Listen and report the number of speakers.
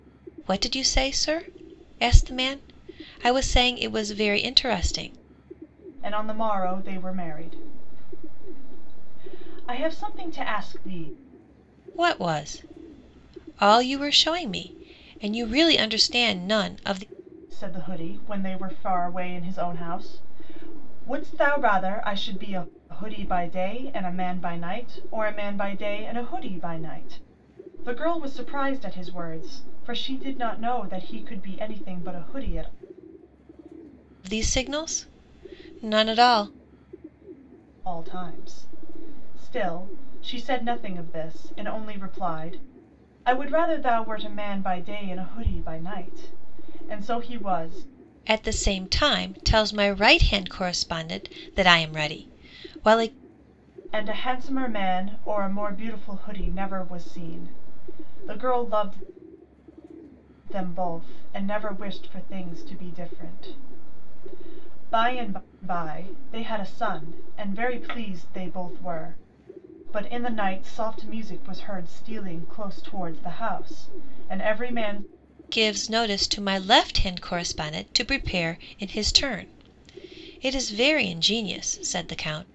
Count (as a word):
two